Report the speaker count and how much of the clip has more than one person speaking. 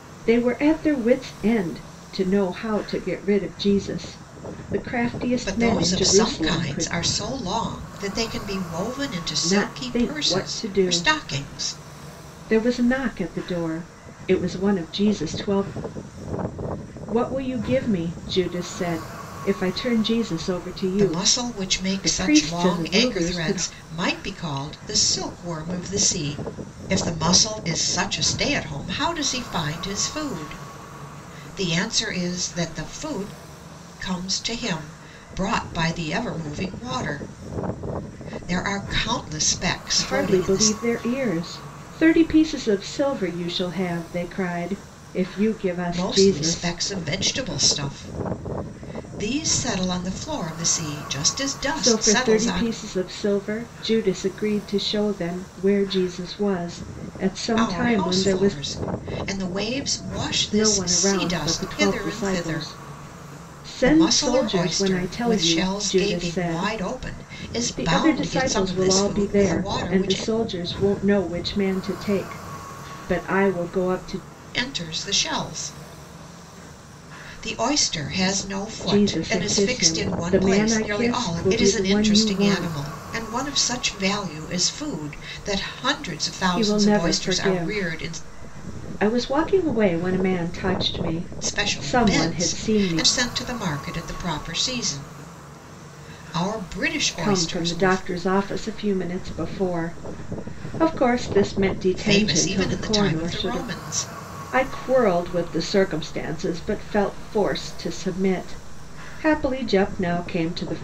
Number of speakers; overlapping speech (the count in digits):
2, about 25%